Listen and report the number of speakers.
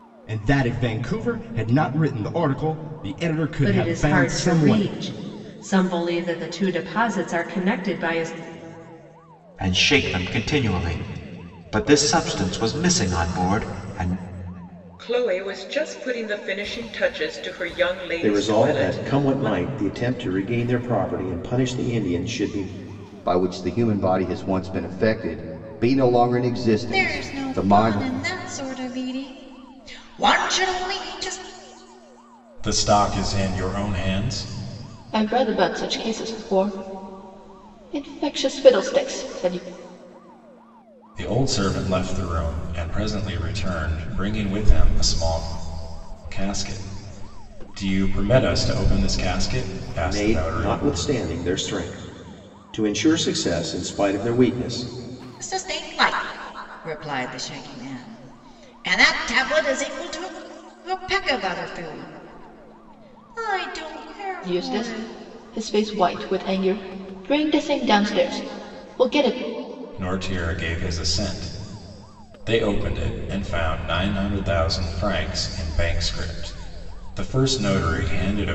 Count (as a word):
nine